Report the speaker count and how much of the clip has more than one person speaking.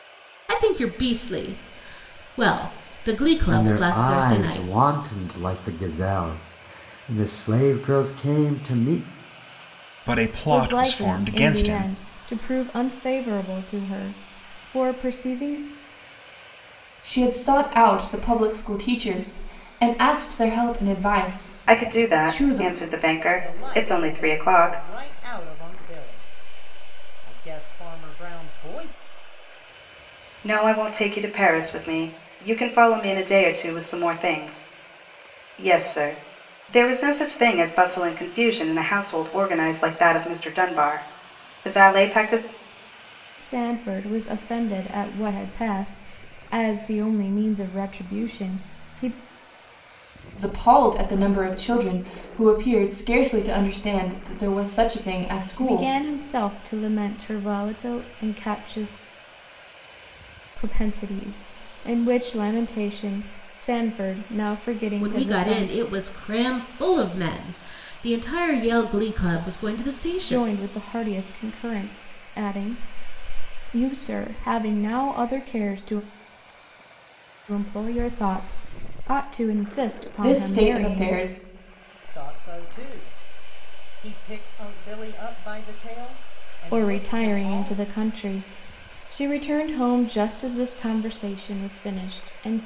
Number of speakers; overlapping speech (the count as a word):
seven, about 10%